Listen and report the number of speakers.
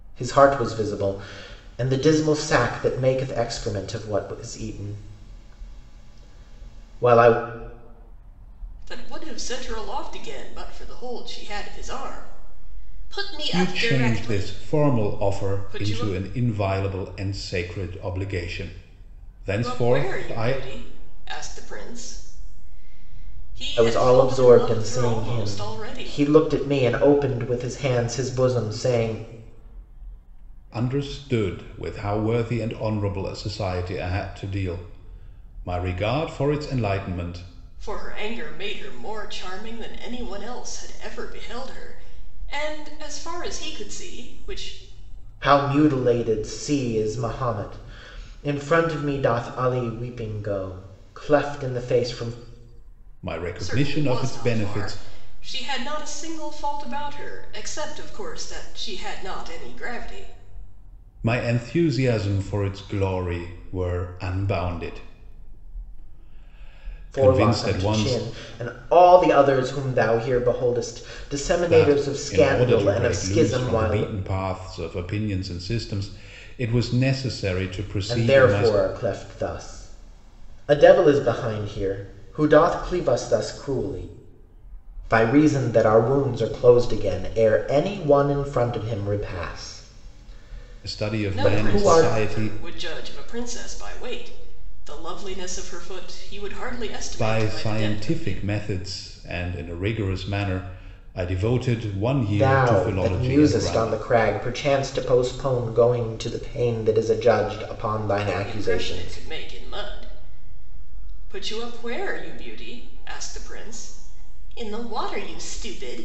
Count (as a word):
three